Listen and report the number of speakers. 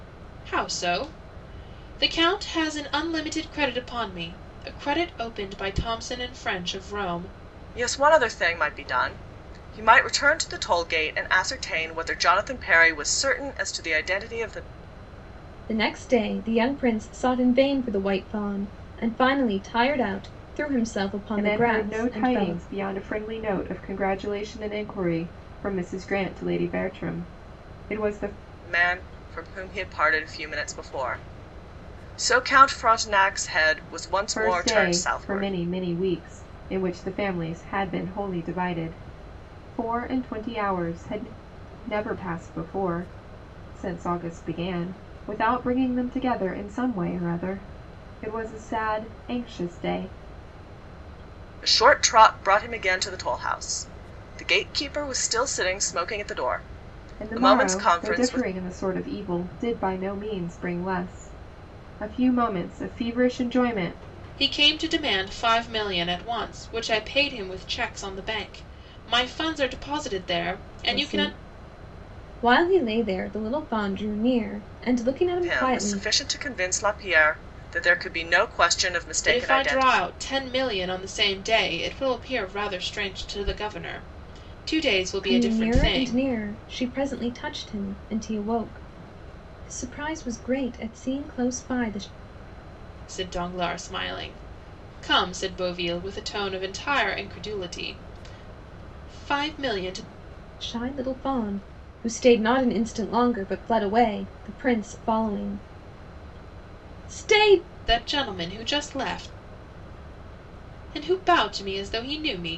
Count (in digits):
4